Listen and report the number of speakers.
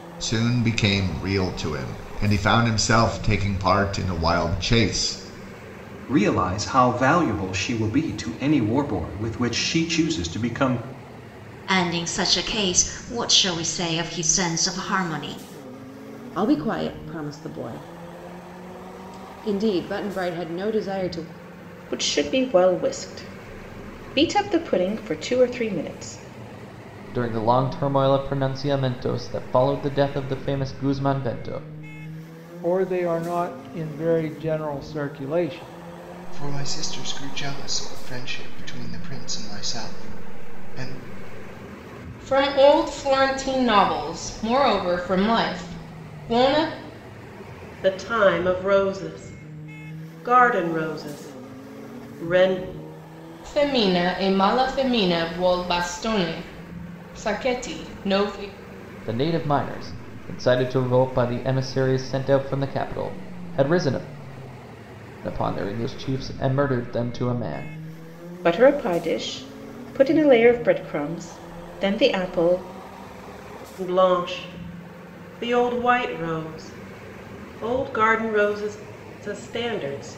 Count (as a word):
ten